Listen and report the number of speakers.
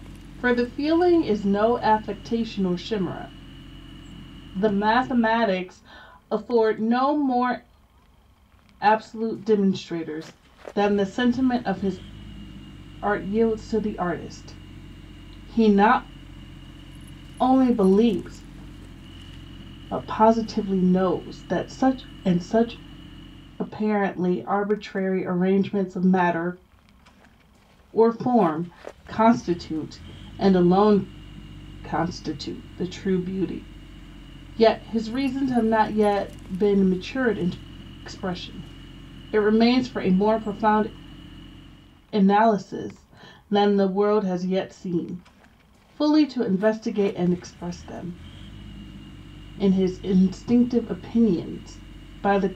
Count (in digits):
1